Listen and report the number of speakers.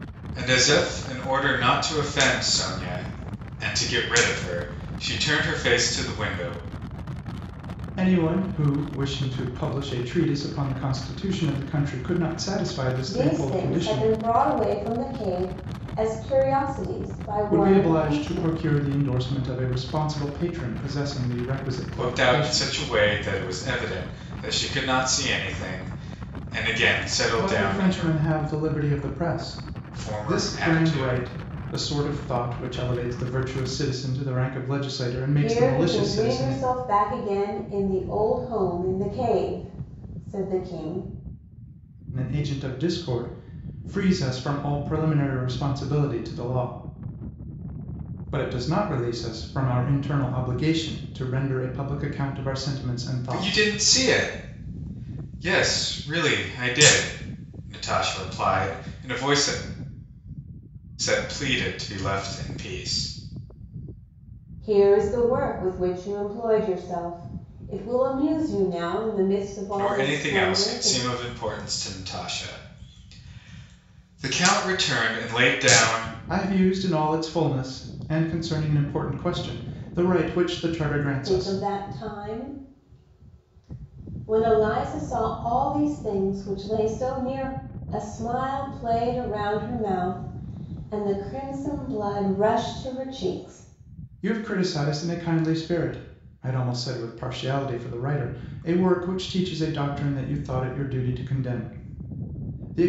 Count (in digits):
3